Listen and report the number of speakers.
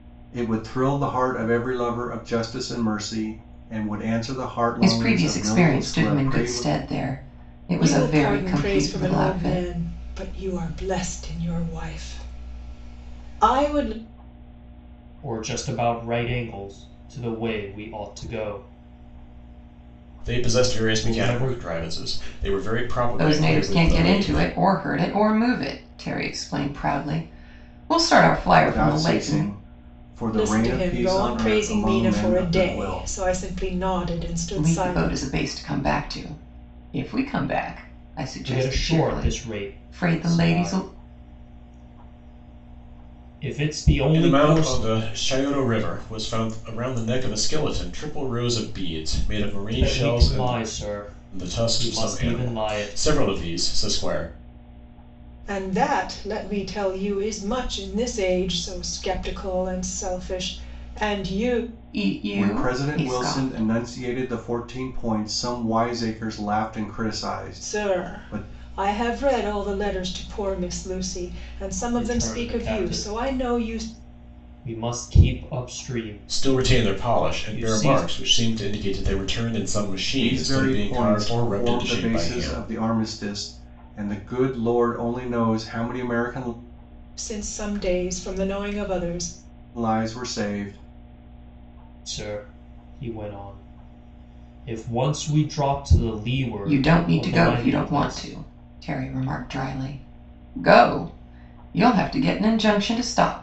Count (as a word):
five